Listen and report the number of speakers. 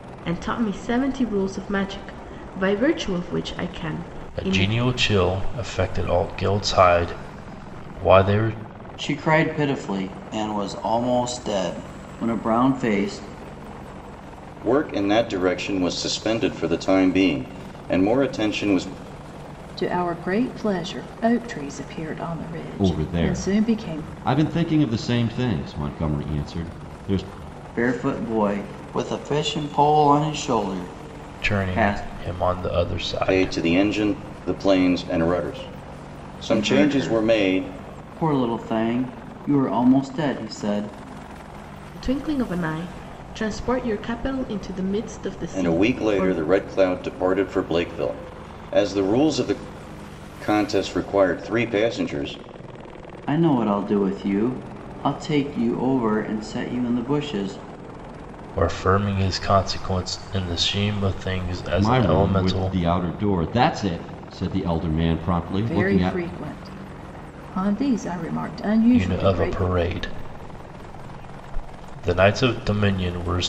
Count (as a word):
six